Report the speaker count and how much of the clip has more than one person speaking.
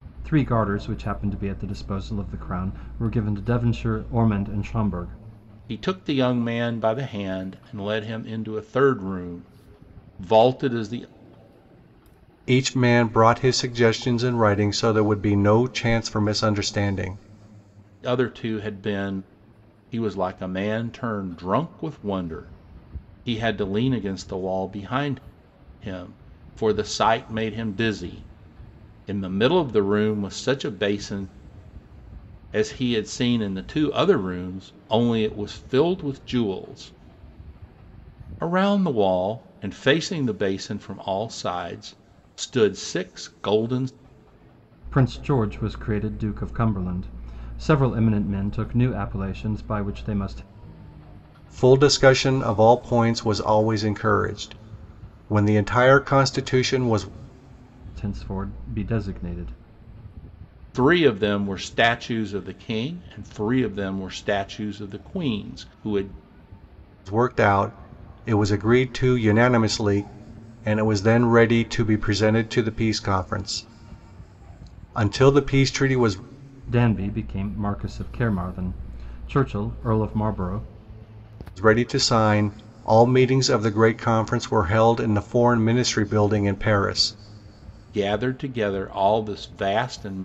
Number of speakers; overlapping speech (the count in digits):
3, no overlap